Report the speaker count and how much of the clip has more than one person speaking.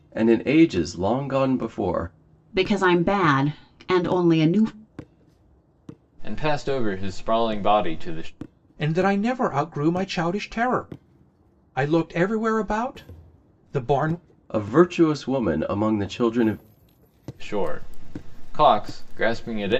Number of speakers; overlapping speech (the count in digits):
4, no overlap